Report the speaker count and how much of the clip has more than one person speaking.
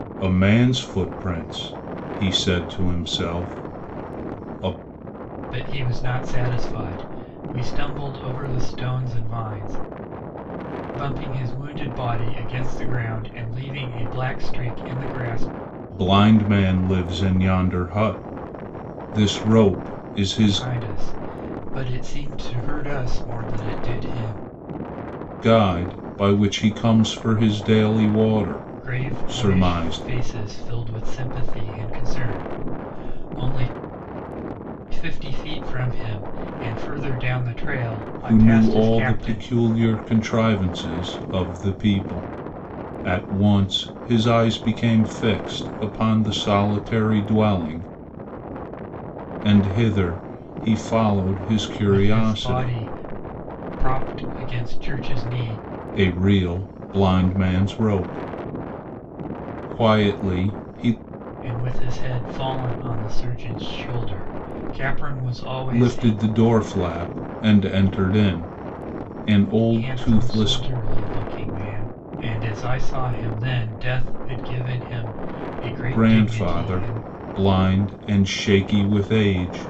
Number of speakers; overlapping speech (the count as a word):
two, about 8%